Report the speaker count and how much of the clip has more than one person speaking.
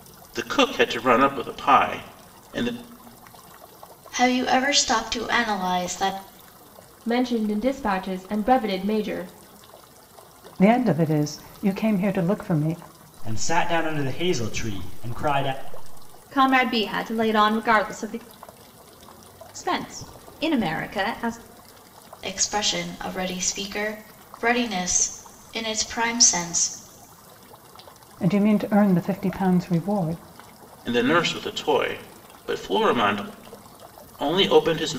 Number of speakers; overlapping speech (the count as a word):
six, no overlap